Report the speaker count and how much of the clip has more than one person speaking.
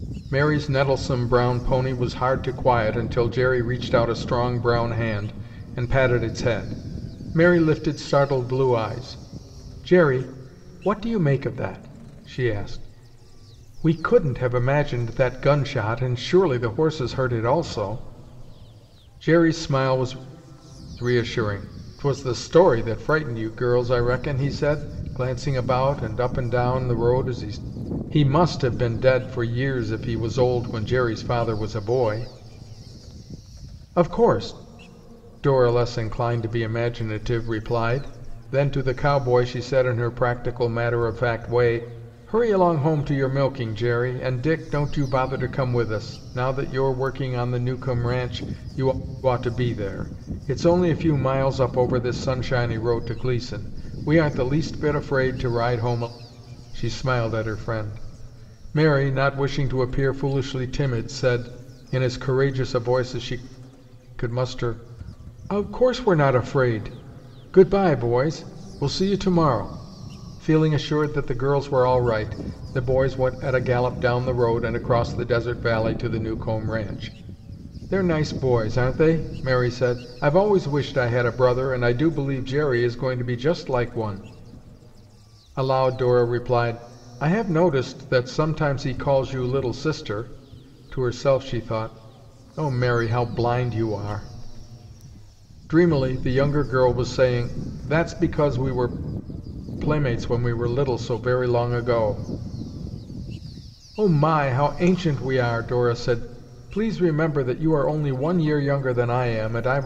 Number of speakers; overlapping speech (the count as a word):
one, no overlap